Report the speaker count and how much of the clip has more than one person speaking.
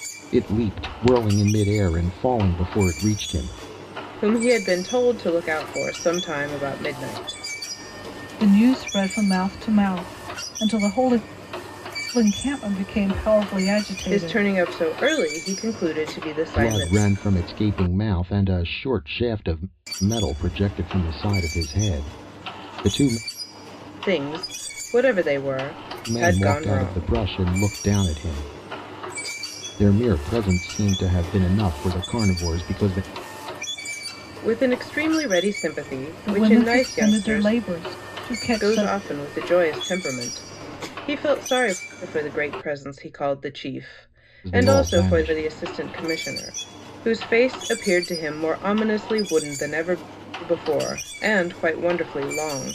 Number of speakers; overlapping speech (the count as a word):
three, about 9%